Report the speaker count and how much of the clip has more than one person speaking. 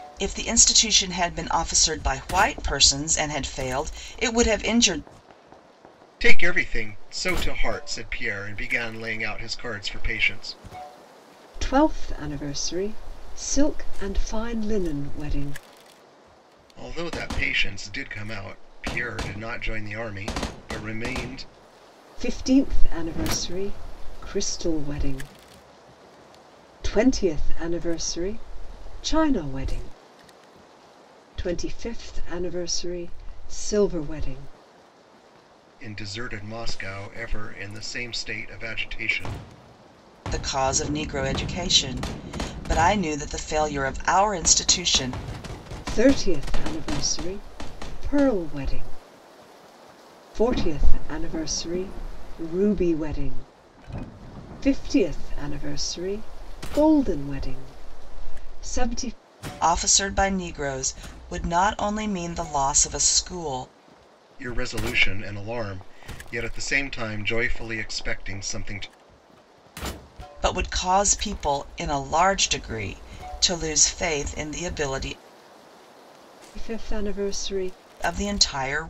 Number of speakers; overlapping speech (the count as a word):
three, no overlap